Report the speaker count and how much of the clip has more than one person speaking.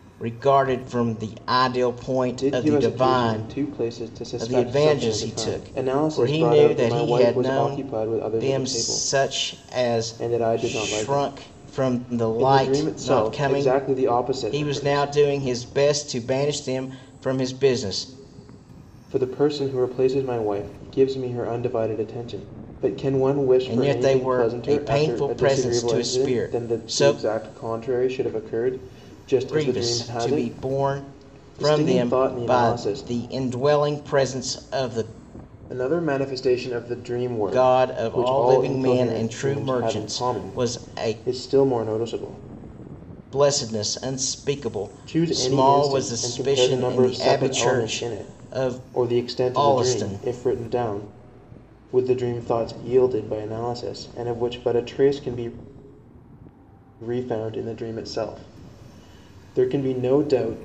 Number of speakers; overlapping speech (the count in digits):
2, about 41%